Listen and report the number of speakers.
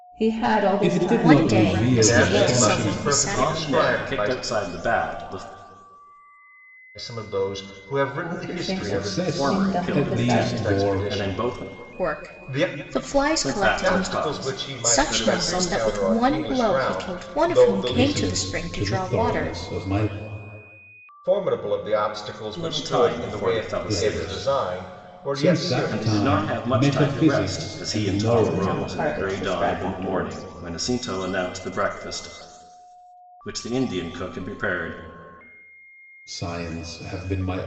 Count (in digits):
5